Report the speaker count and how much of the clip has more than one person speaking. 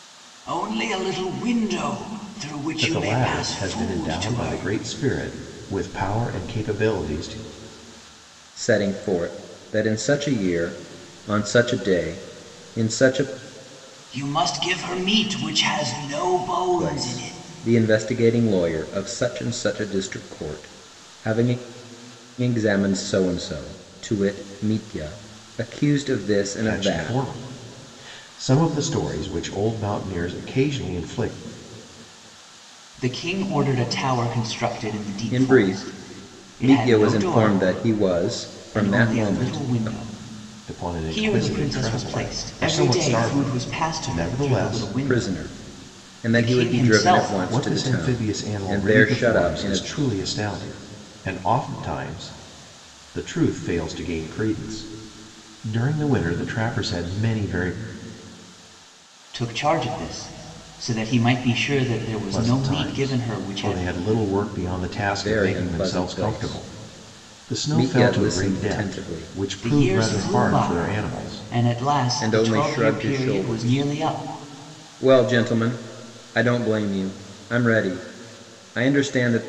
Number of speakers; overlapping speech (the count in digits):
3, about 32%